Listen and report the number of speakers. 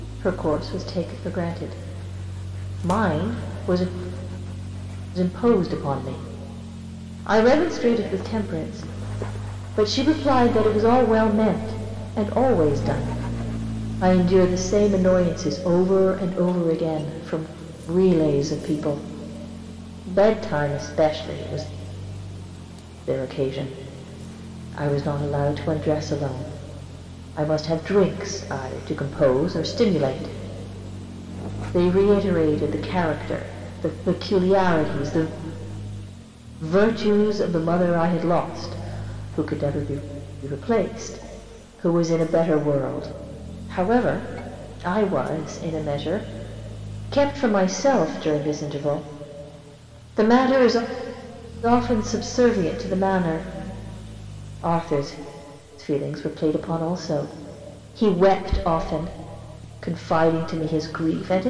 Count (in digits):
1